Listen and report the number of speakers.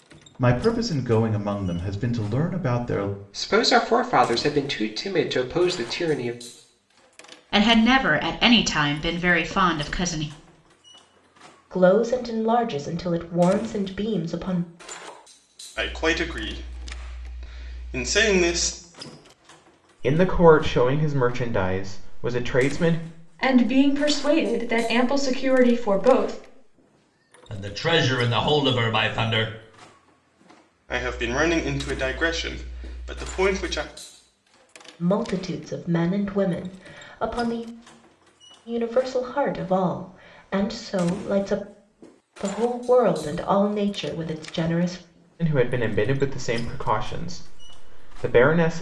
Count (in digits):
8